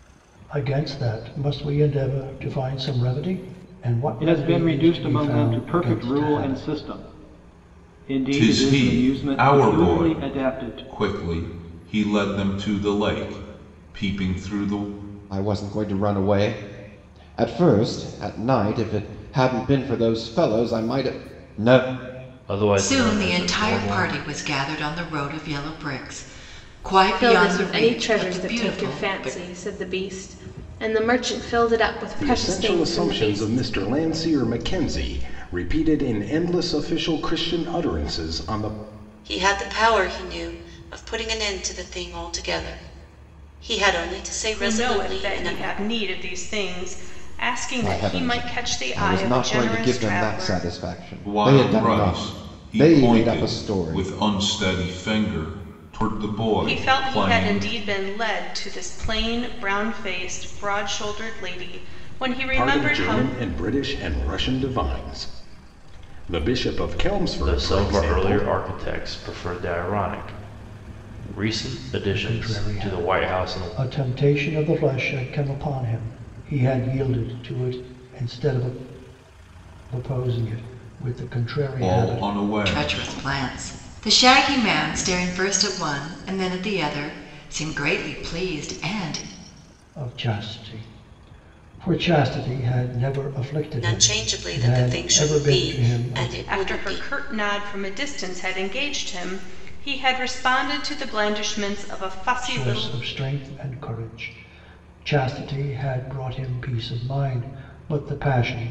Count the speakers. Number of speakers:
10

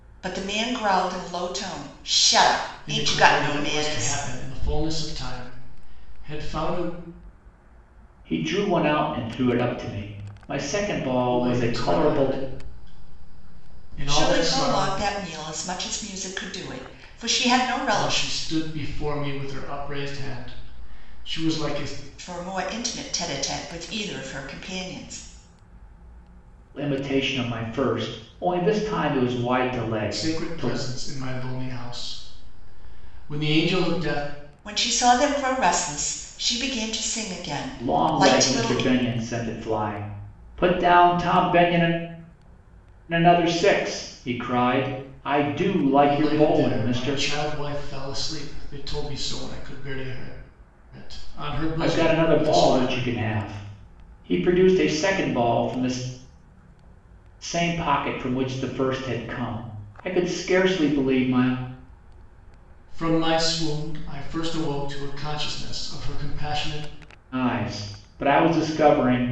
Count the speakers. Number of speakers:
3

